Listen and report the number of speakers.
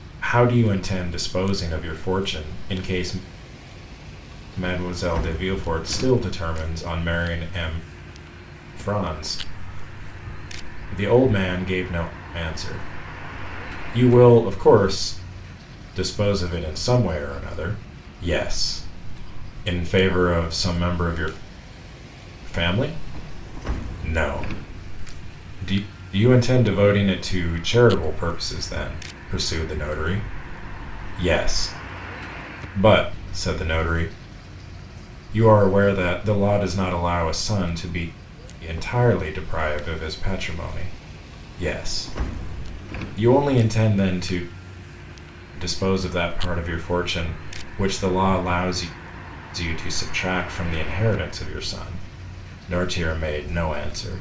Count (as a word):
one